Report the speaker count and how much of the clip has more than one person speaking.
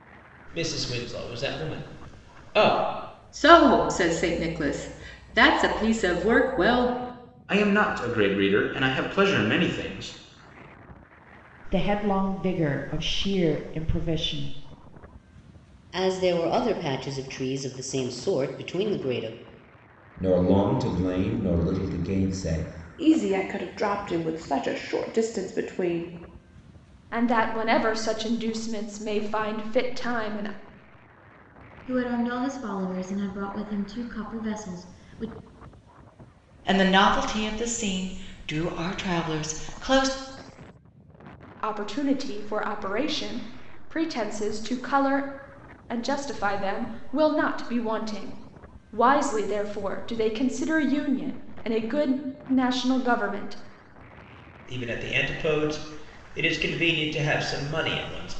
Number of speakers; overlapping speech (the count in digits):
10, no overlap